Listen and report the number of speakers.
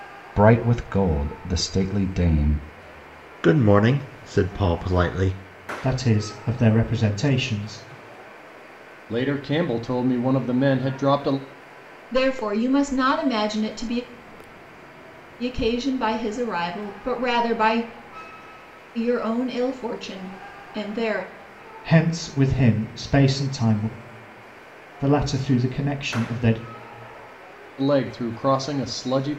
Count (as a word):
five